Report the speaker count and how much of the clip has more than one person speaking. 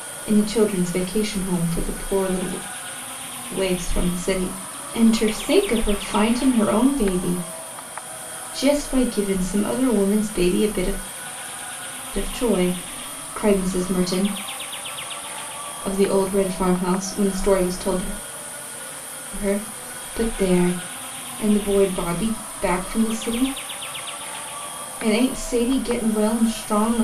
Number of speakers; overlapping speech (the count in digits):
1, no overlap